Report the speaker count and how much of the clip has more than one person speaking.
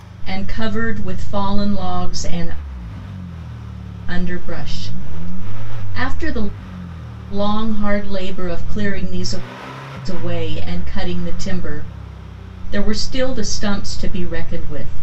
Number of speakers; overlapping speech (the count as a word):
one, no overlap